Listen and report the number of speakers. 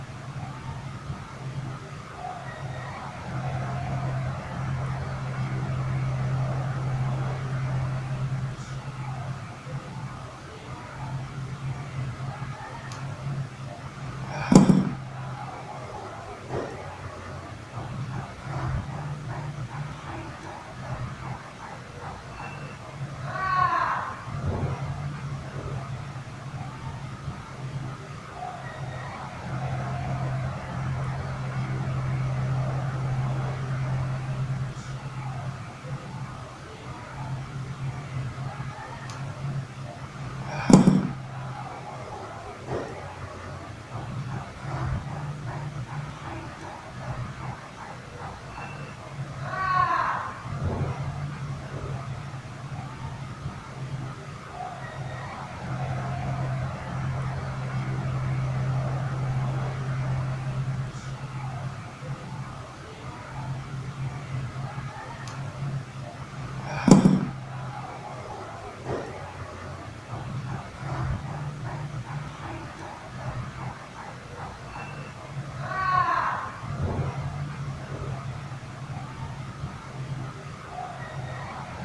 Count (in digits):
0